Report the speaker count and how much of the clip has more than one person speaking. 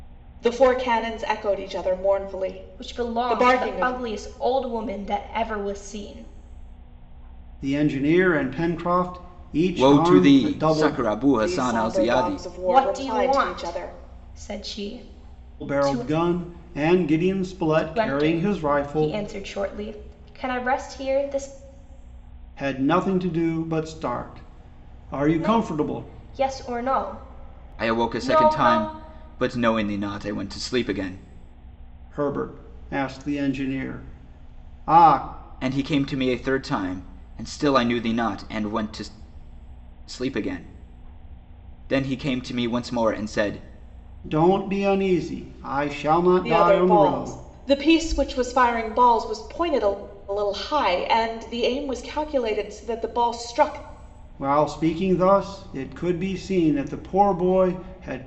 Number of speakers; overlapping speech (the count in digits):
4, about 16%